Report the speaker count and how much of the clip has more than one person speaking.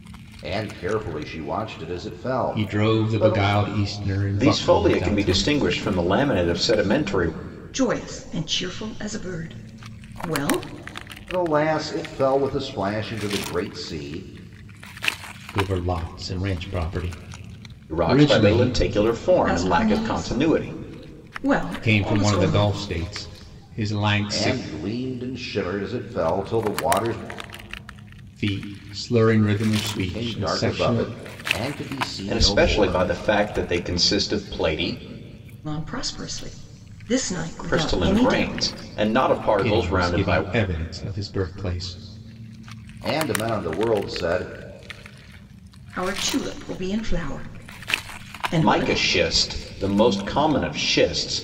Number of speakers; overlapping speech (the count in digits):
4, about 20%